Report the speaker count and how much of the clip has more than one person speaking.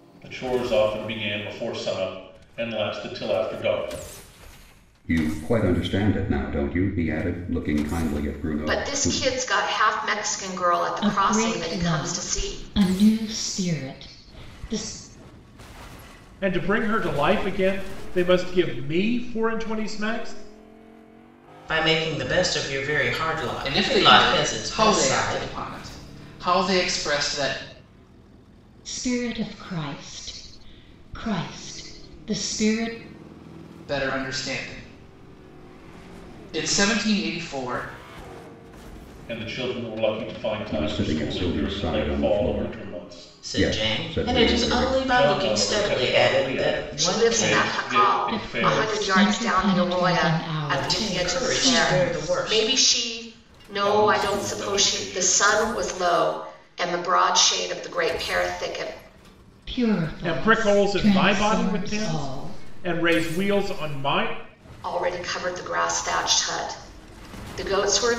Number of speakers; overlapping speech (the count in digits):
7, about 29%